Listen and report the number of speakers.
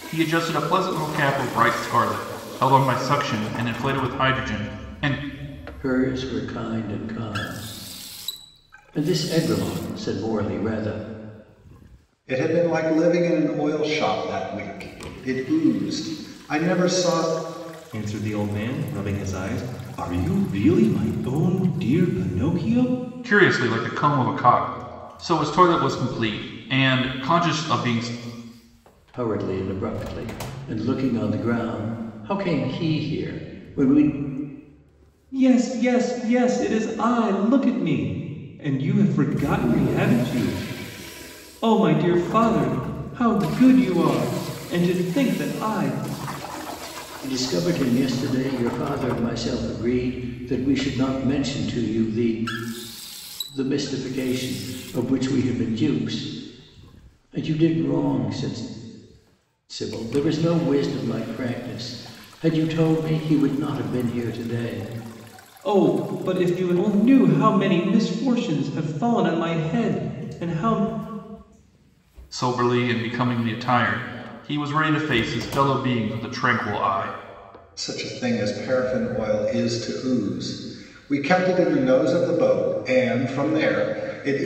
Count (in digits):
4